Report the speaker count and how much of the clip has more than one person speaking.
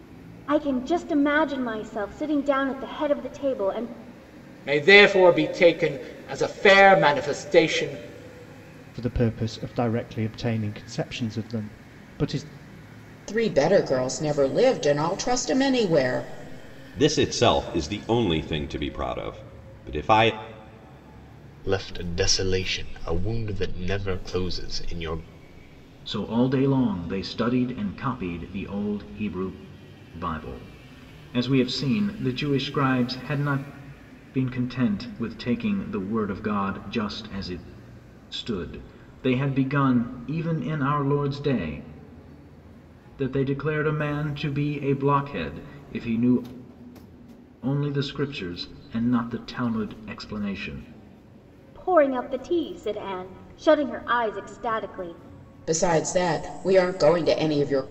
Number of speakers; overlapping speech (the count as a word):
seven, no overlap